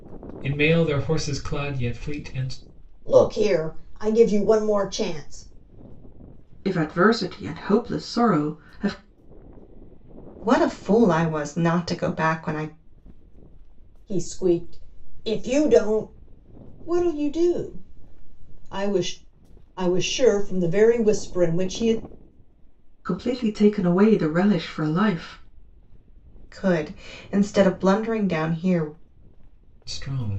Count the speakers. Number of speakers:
4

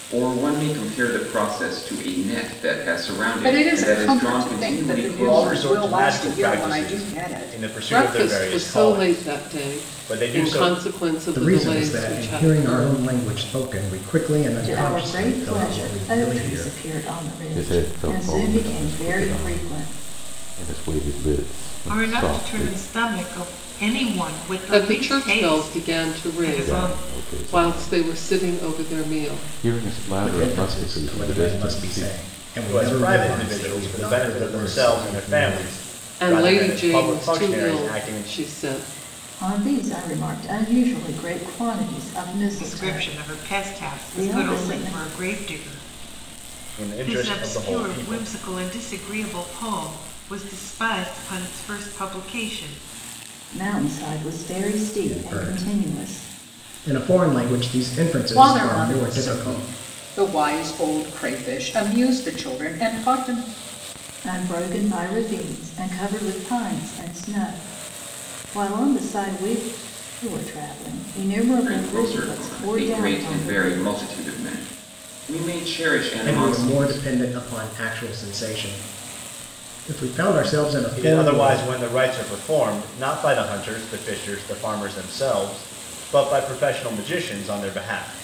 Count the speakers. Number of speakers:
8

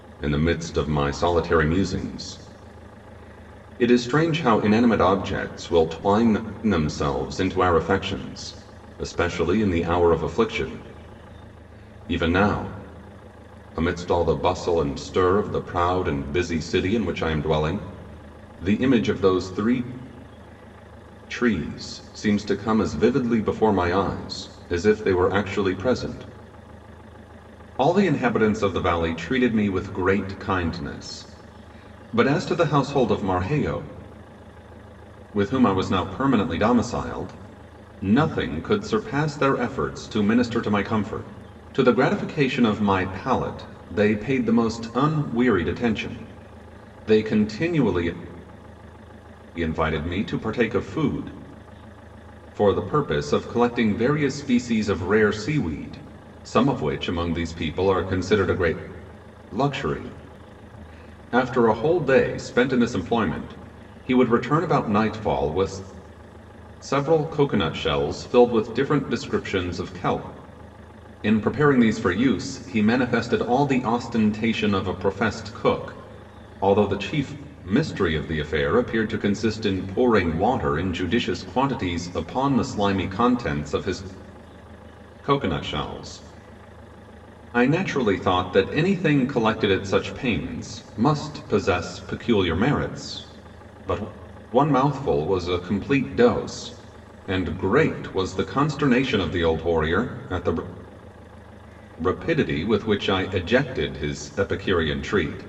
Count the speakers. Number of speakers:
1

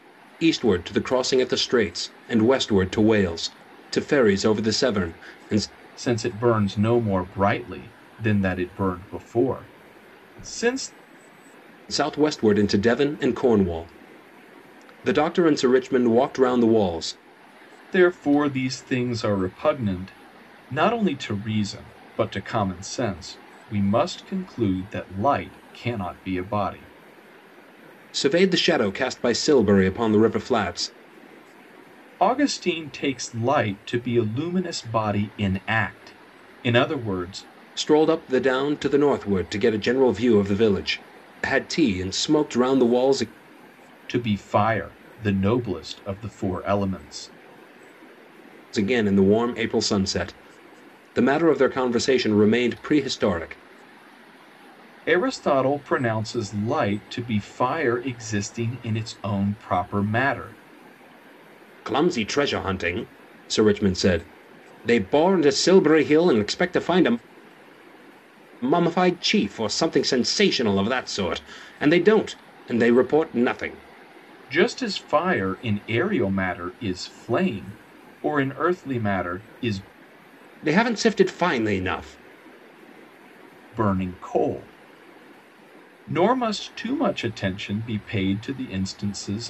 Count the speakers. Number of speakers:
2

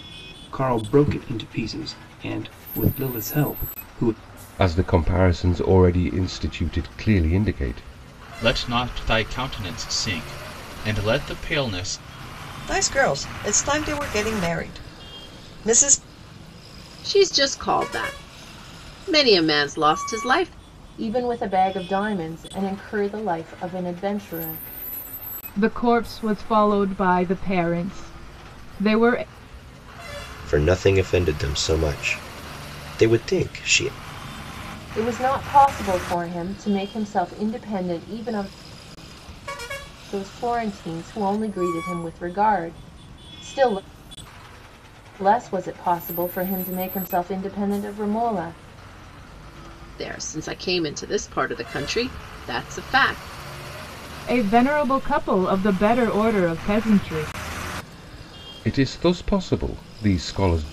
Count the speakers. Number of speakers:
8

